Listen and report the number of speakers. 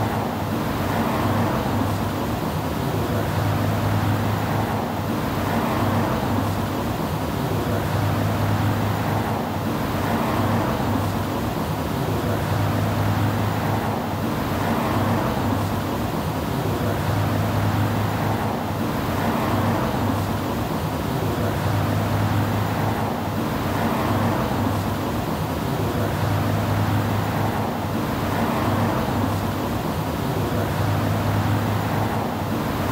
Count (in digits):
0